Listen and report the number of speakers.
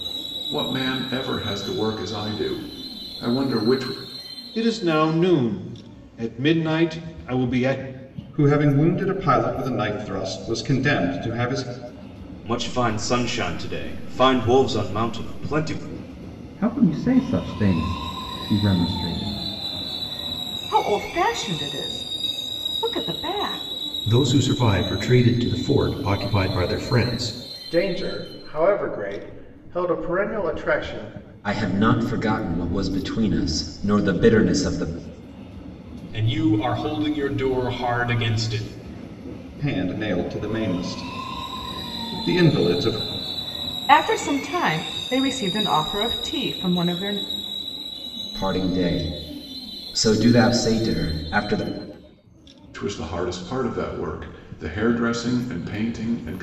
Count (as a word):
ten